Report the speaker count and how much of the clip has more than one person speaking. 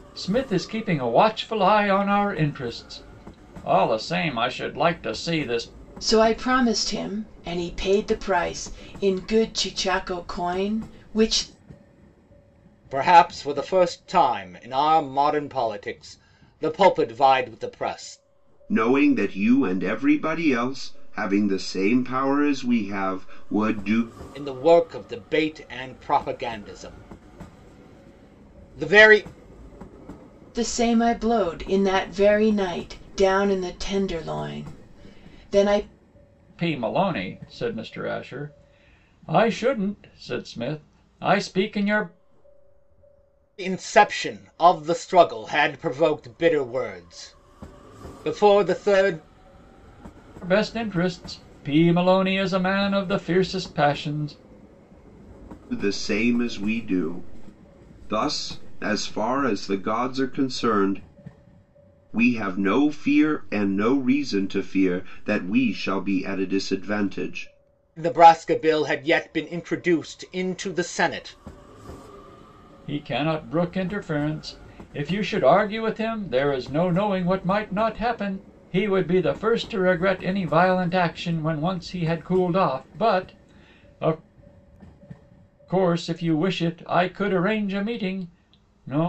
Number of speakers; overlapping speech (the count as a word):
four, no overlap